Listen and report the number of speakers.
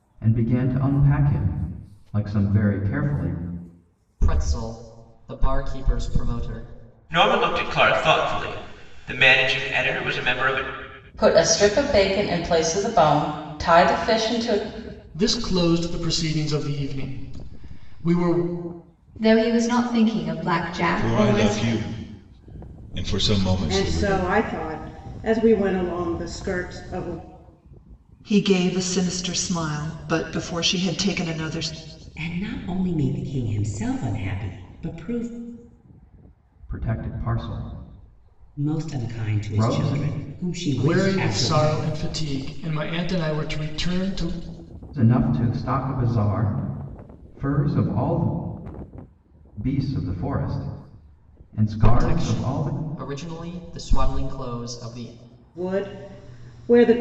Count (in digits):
10